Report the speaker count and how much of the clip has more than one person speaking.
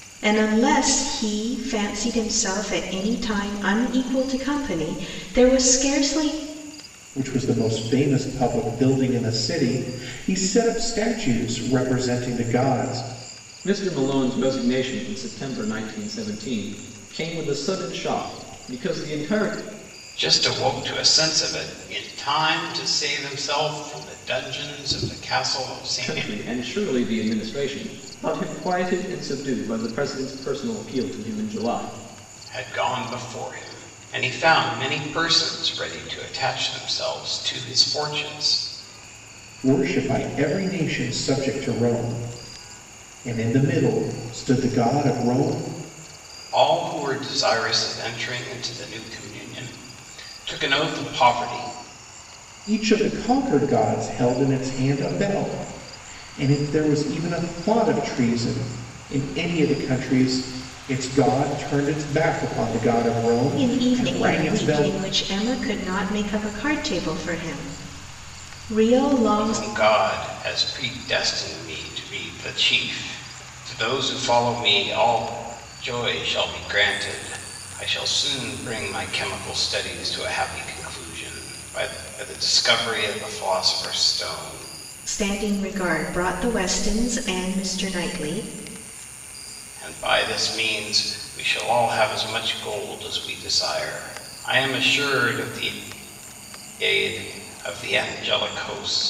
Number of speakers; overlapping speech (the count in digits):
4, about 2%